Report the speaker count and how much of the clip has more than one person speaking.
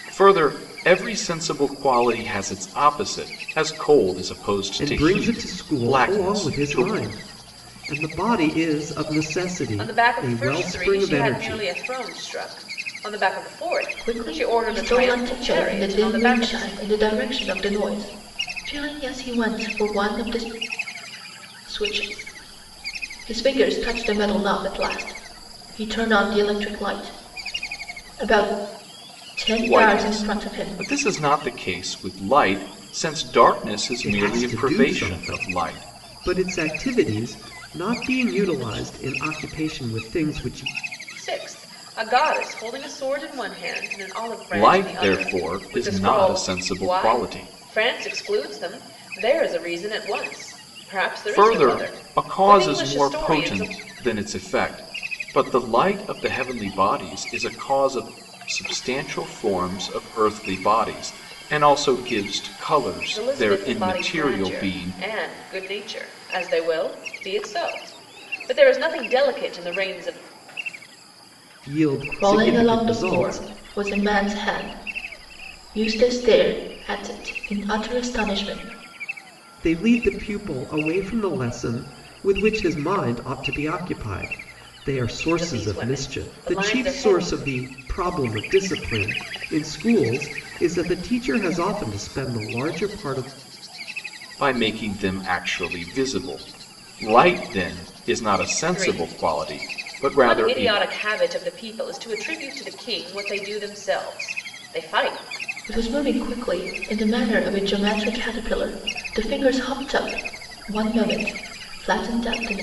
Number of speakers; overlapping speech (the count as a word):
four, about 20%